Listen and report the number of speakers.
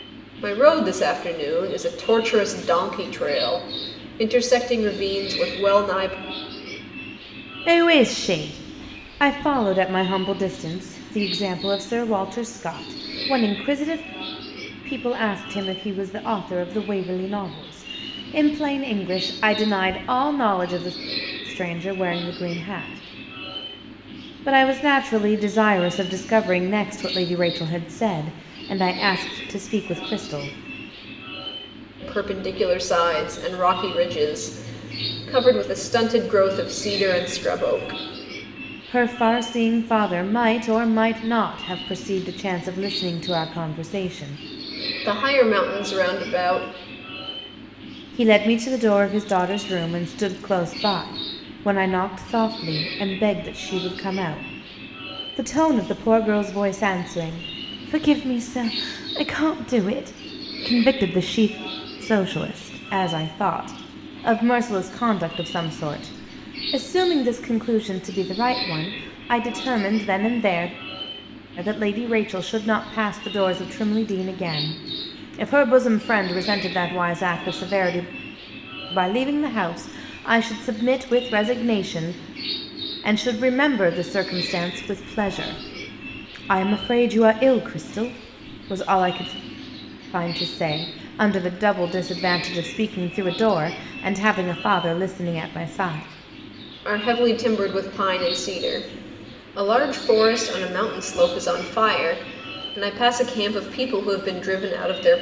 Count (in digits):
2